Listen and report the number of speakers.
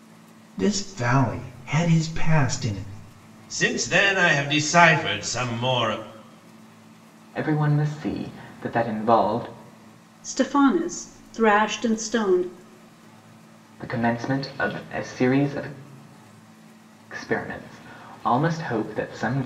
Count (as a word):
four